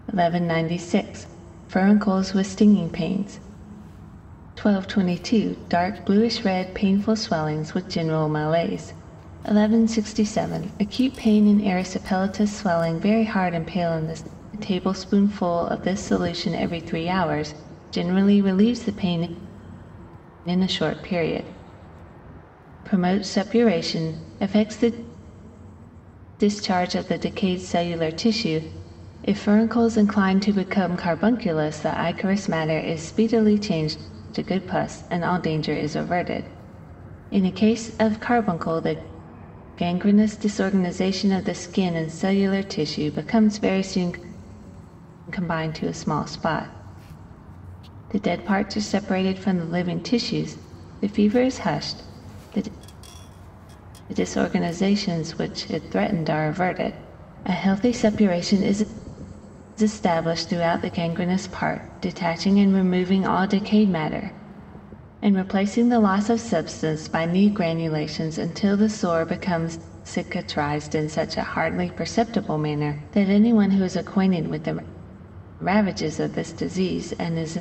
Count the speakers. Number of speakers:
one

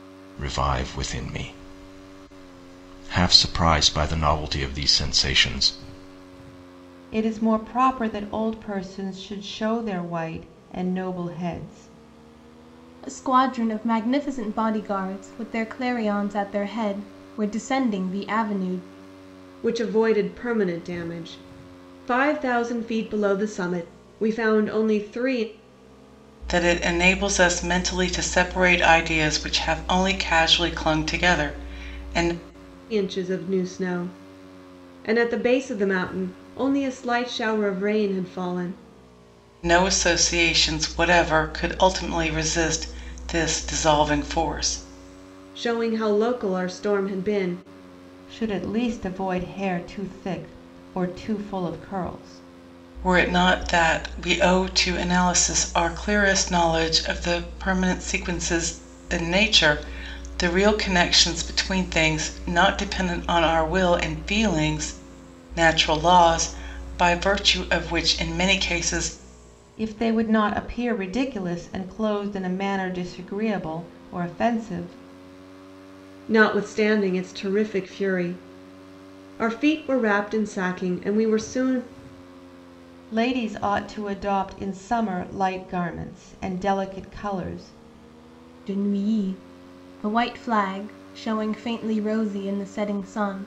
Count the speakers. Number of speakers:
five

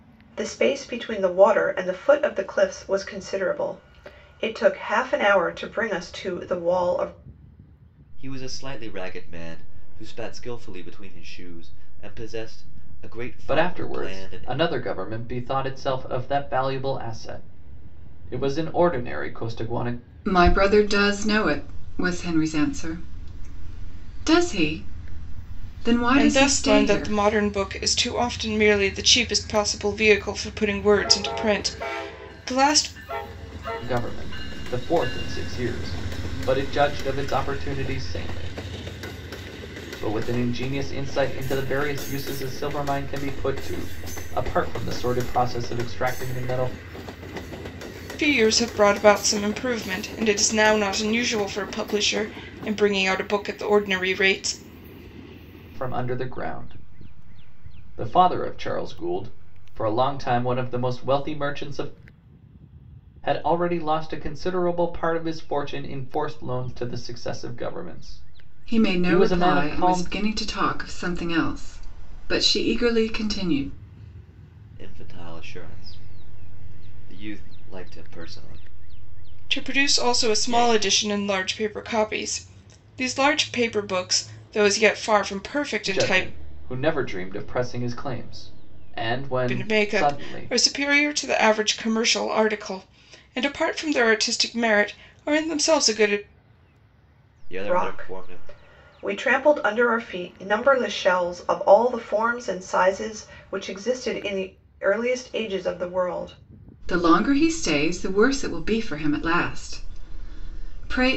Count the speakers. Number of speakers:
five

